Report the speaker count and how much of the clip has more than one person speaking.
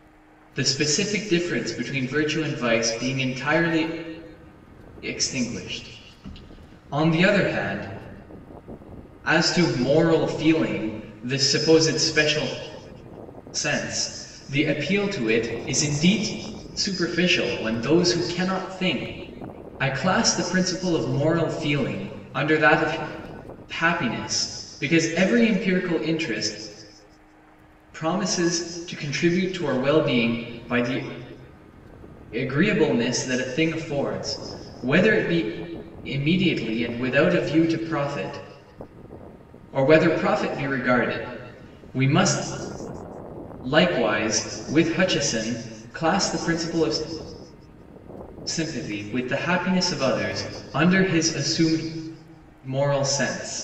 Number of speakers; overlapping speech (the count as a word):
one, no overlap